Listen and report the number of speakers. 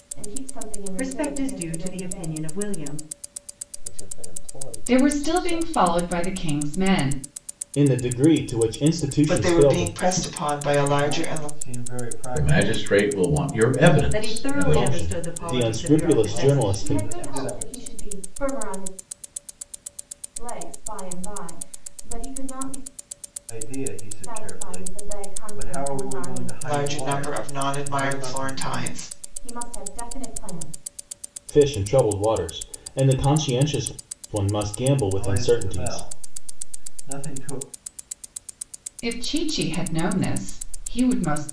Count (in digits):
8